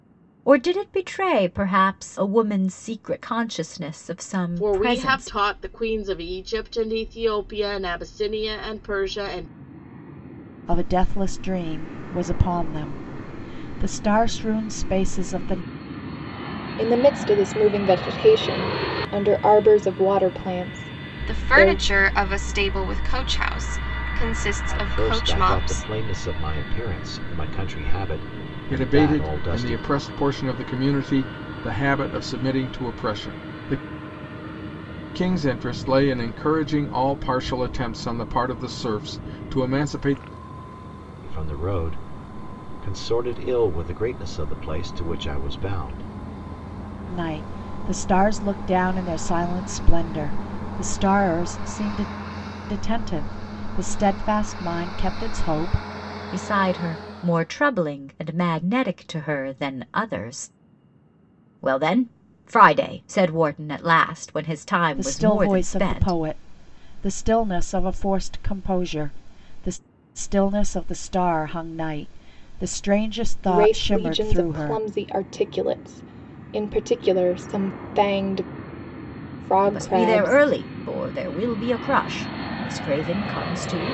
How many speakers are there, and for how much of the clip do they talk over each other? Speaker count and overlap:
seven, about 9%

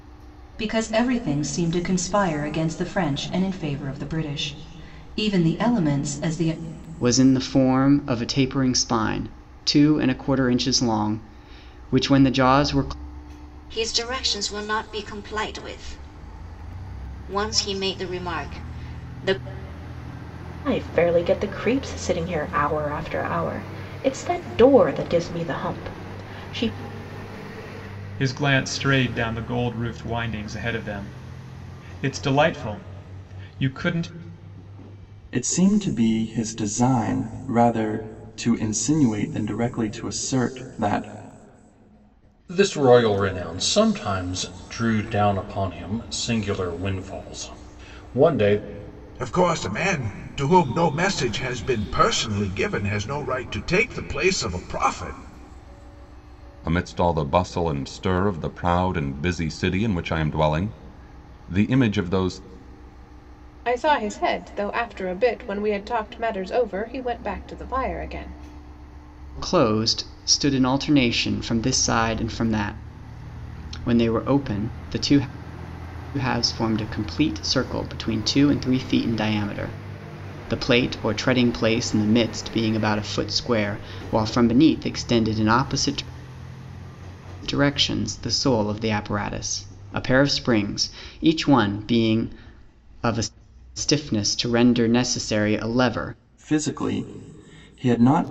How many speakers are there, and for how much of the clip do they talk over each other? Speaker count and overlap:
ten, no overlap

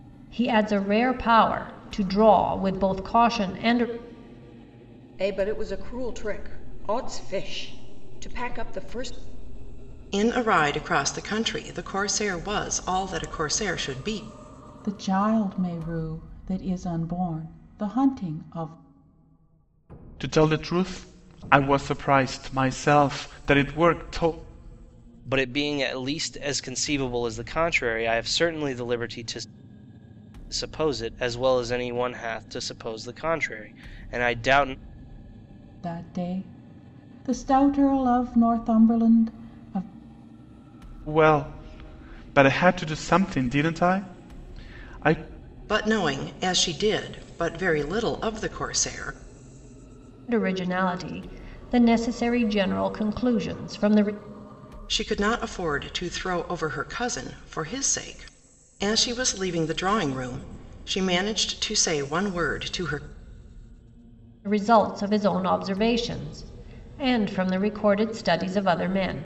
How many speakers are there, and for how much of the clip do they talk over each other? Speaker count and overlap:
six, no overlap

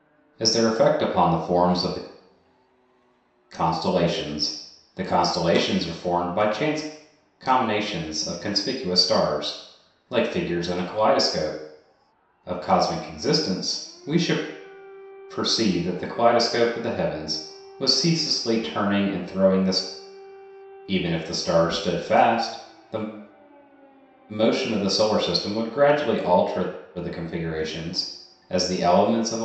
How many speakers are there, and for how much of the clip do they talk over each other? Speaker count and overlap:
one, no overlap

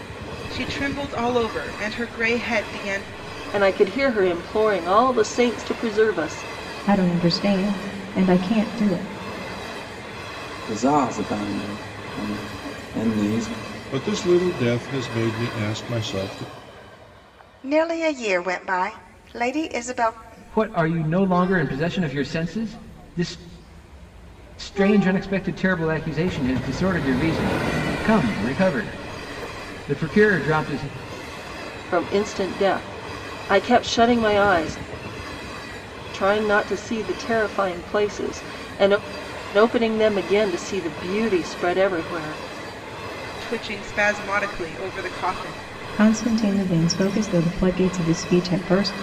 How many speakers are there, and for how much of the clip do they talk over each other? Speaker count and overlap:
seven, no overlap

